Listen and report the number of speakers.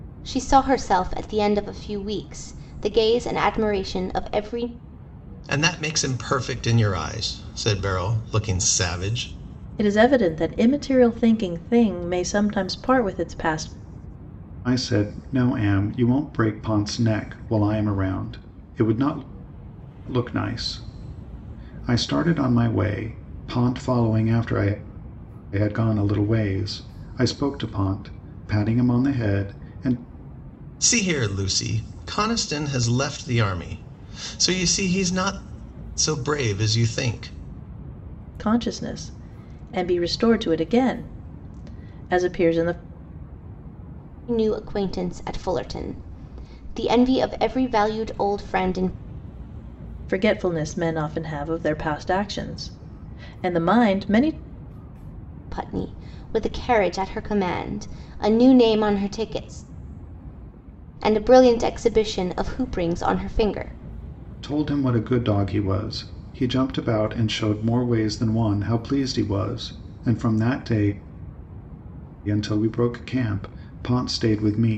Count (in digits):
4